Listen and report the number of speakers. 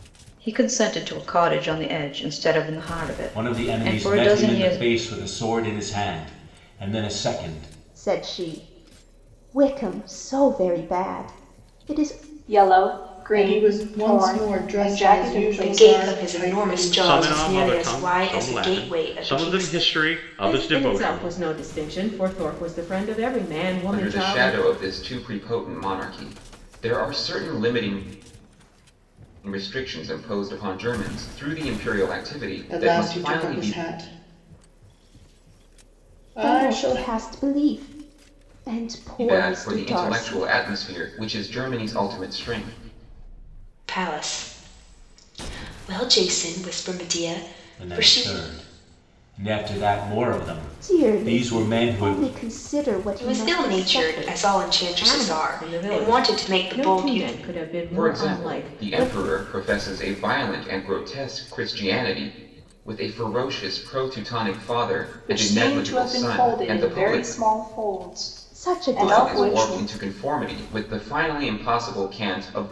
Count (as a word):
nine